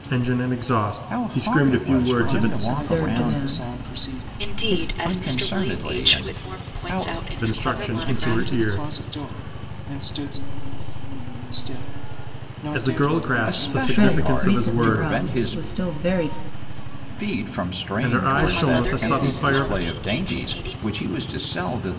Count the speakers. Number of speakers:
5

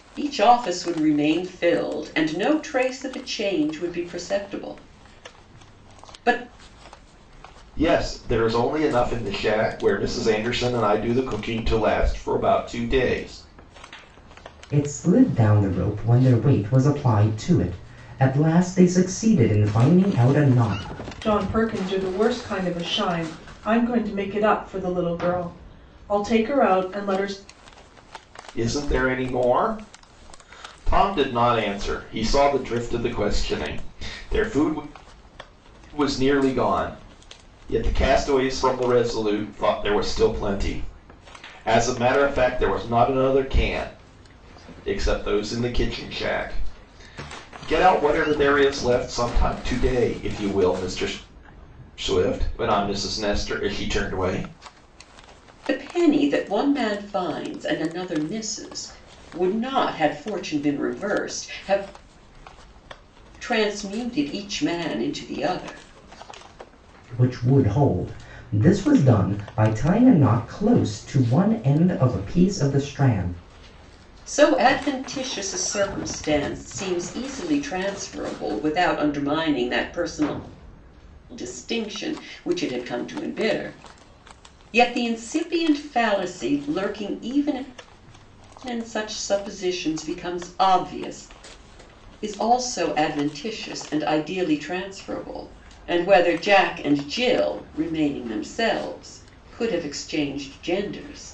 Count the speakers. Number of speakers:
4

